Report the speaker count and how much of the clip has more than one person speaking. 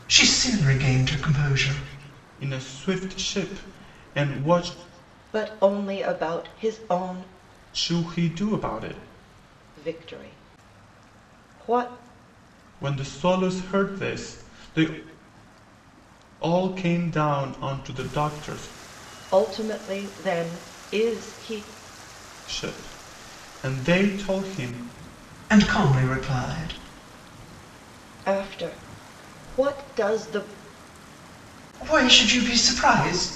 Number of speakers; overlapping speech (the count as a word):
three, no overlap